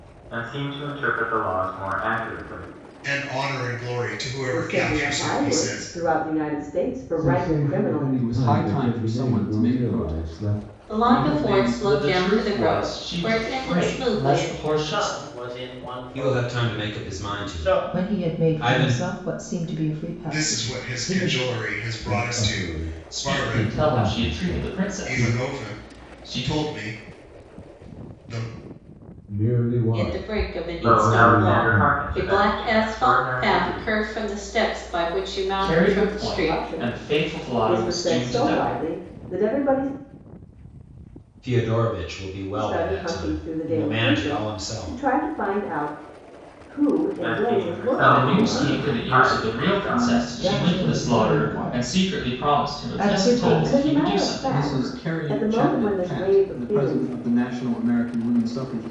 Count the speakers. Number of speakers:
10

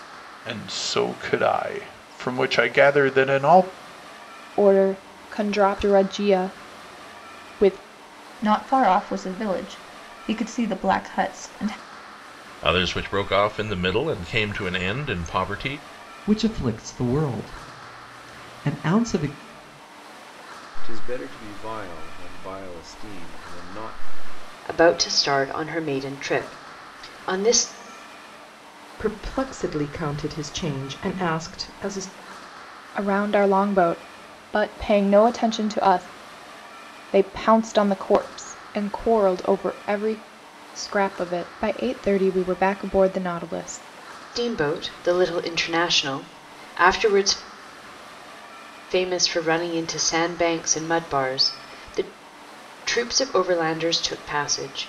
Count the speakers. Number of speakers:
8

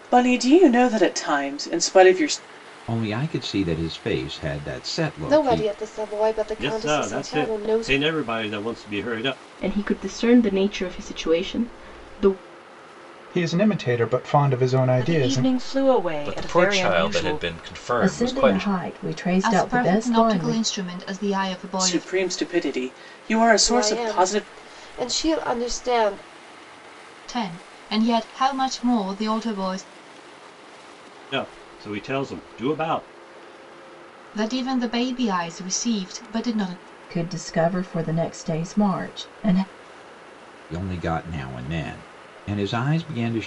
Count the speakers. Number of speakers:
10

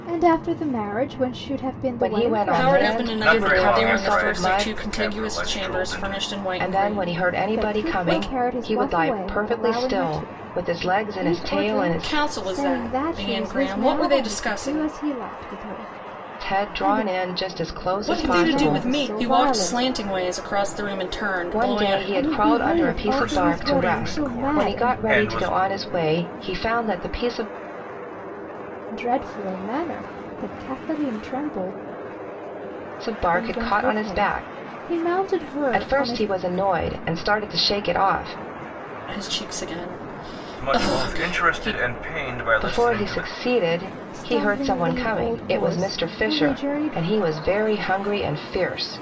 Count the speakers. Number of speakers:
4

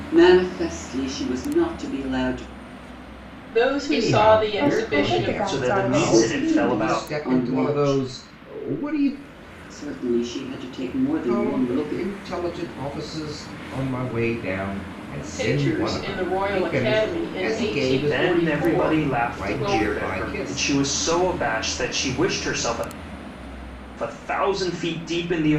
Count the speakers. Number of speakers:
5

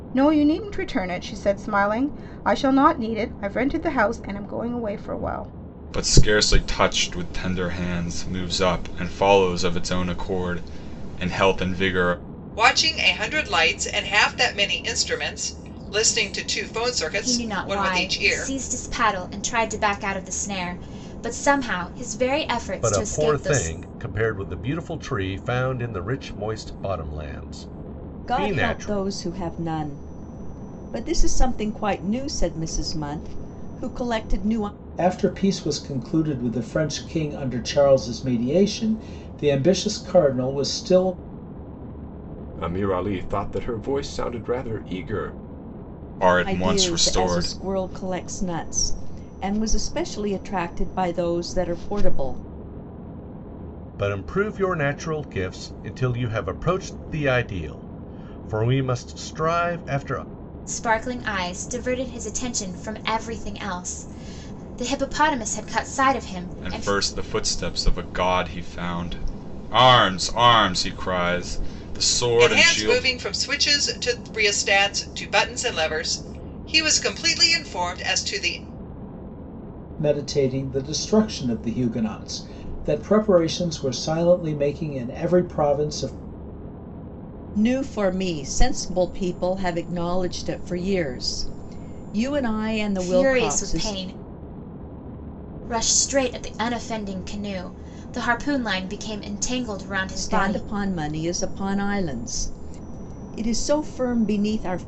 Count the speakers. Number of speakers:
8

